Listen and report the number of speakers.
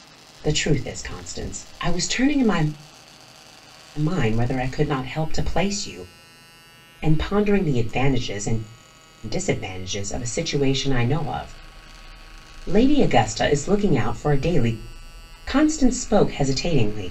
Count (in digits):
1